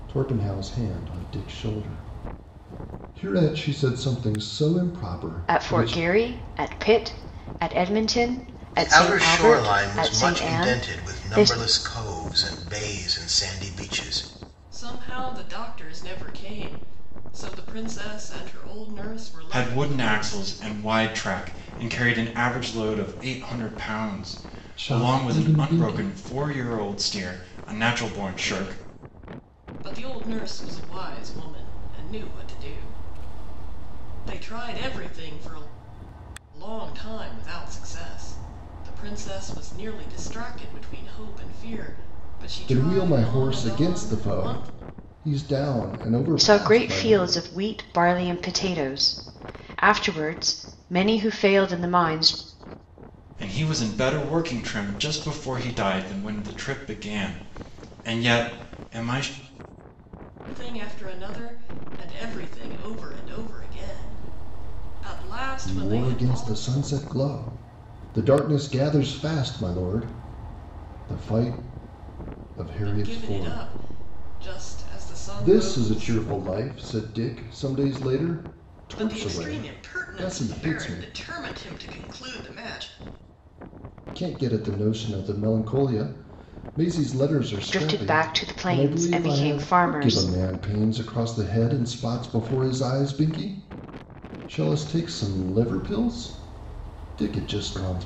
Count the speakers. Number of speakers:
five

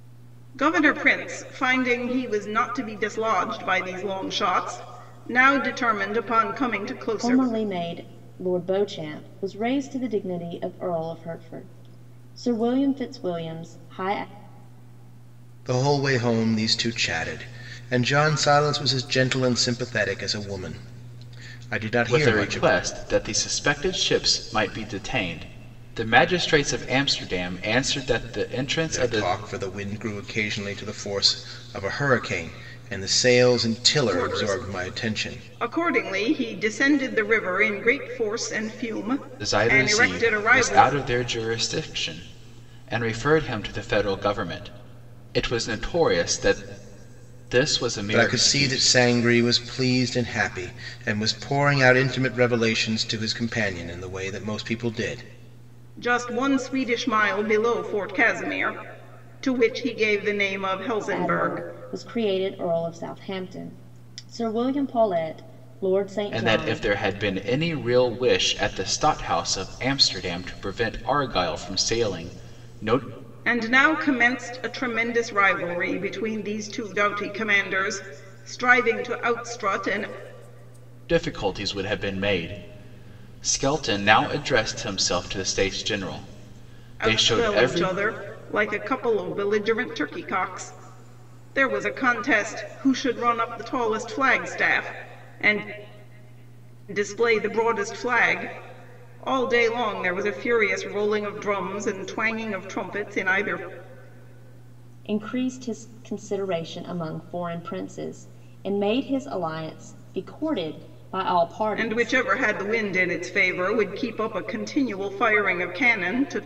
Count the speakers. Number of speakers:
four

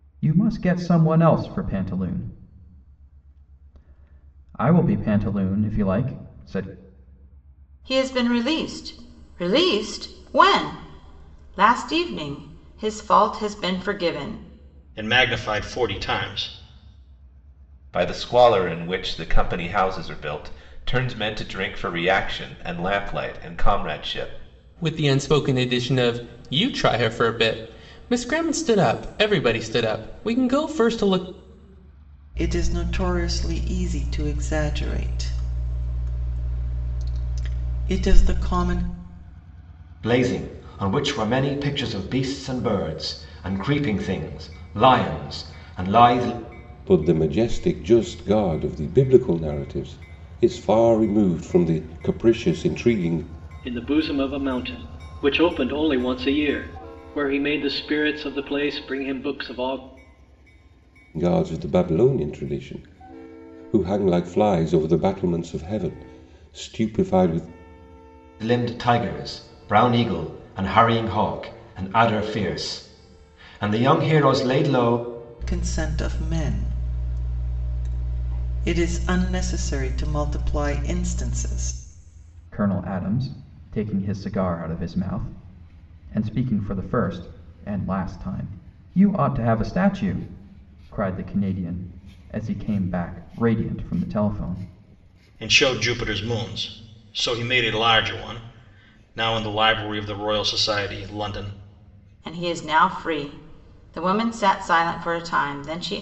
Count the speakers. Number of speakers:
nine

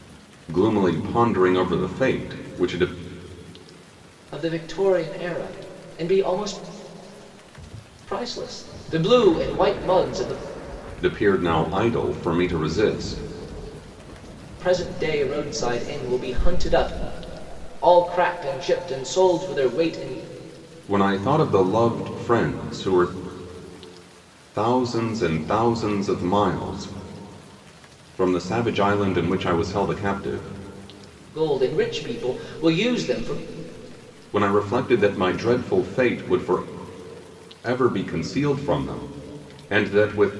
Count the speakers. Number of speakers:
two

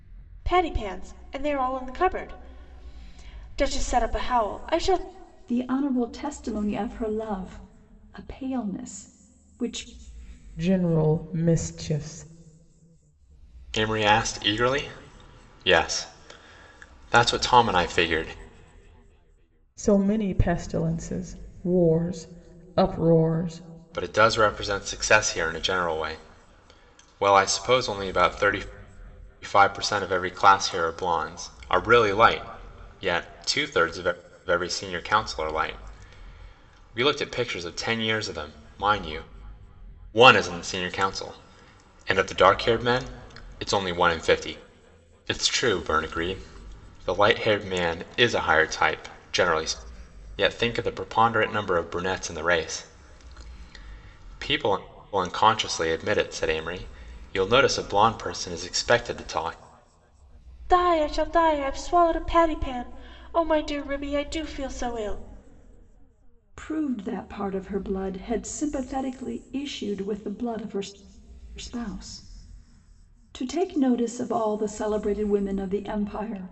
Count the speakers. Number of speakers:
four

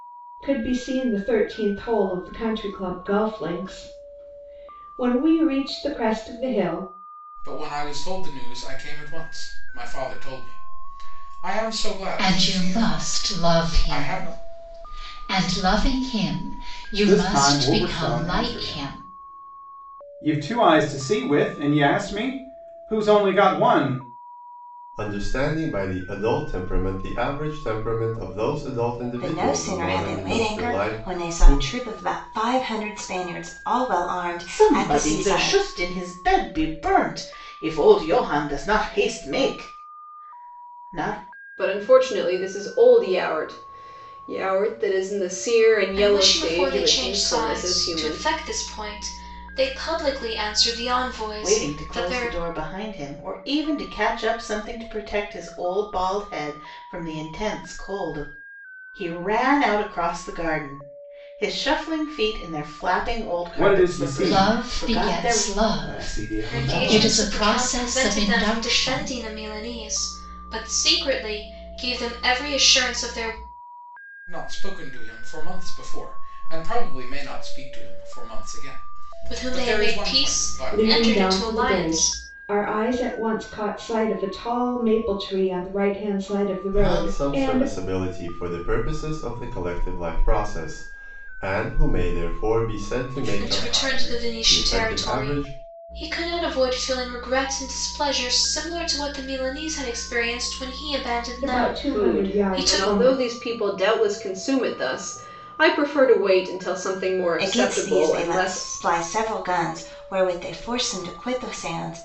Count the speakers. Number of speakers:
nine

